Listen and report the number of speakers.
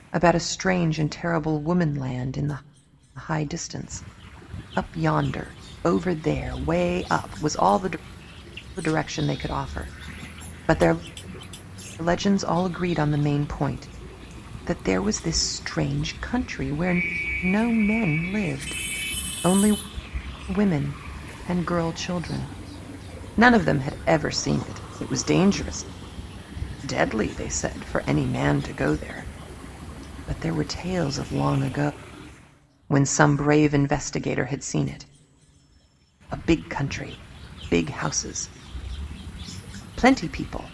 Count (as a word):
one